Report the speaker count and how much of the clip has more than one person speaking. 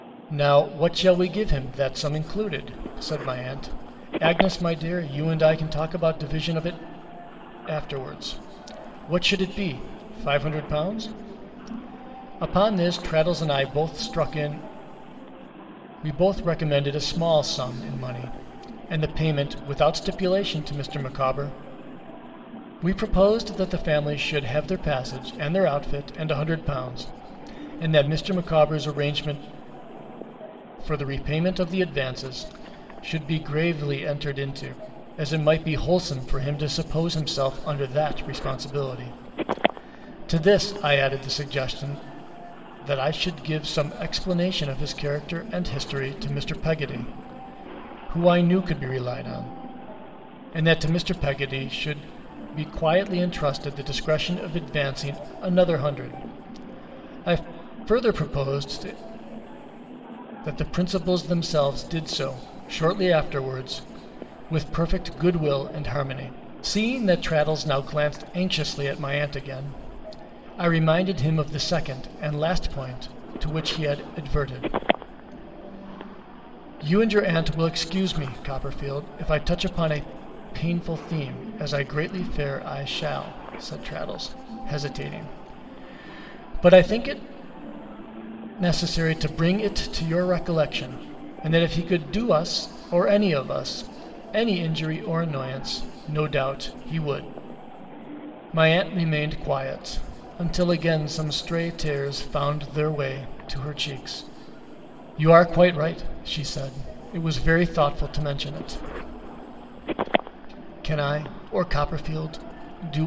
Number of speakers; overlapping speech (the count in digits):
1, no overlap